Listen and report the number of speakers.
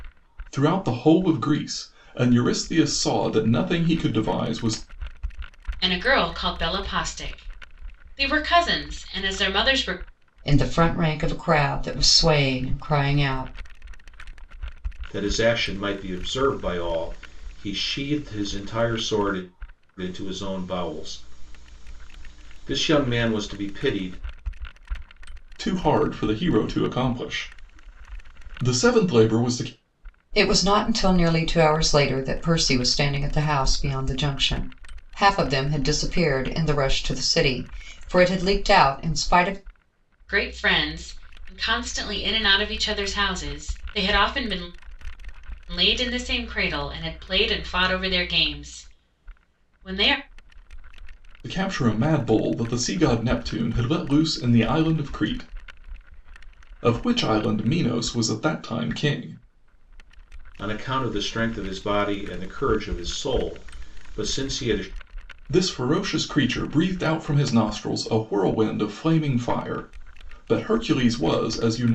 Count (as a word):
four